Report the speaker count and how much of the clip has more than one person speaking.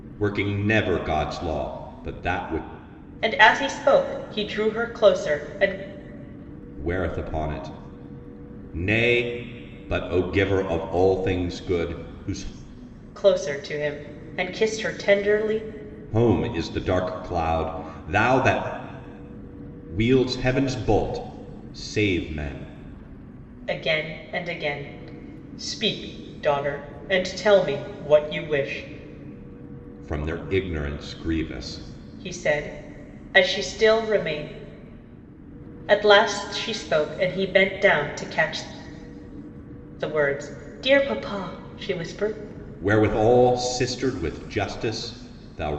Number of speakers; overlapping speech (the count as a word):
two, no overlap